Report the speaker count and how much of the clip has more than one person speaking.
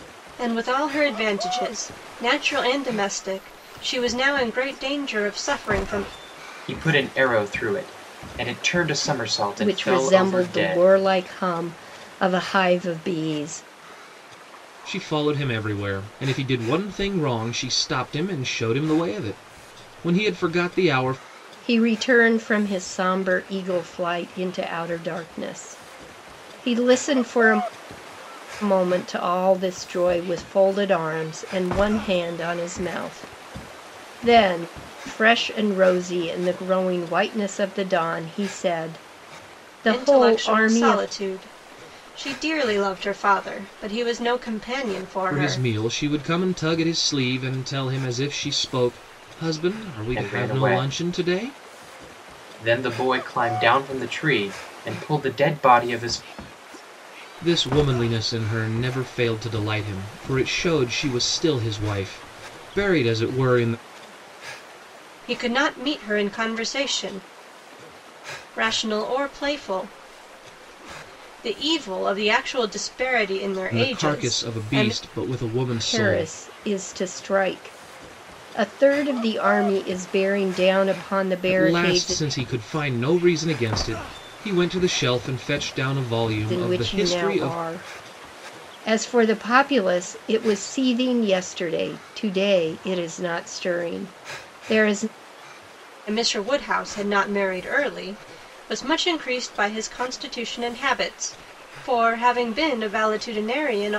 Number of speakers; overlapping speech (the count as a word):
four, about 8%